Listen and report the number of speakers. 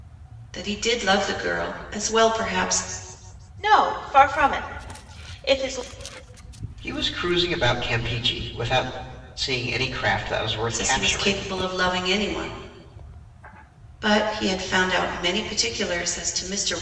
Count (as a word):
three